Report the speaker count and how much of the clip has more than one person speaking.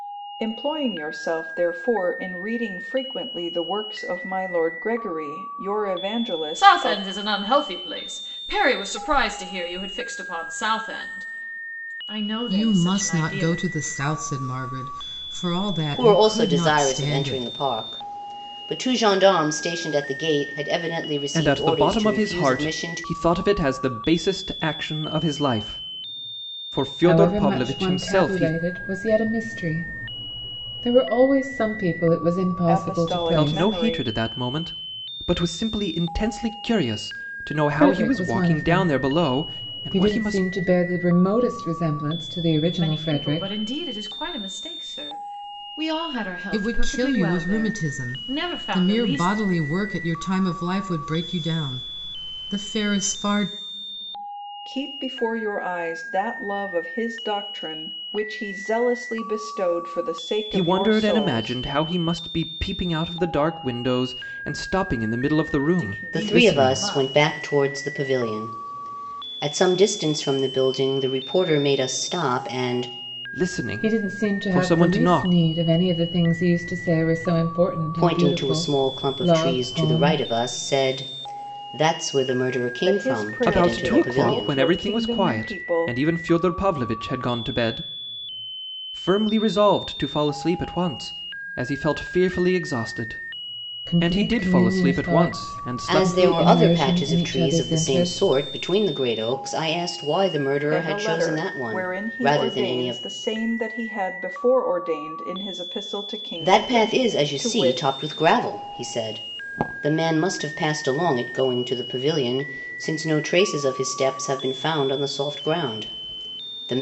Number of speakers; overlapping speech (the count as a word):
six, about 28%